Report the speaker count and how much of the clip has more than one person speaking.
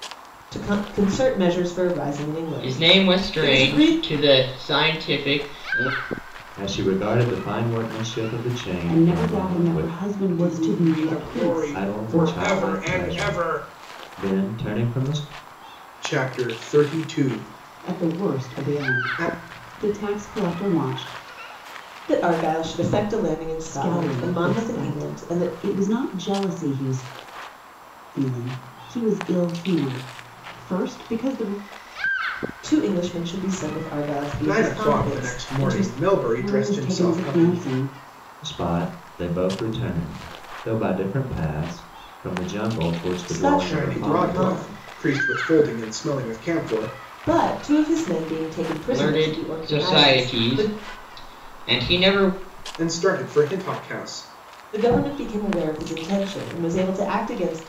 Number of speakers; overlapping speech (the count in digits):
5, about 27%